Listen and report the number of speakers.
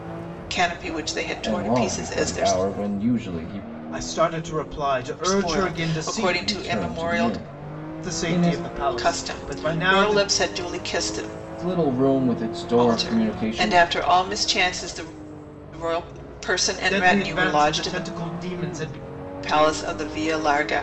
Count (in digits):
3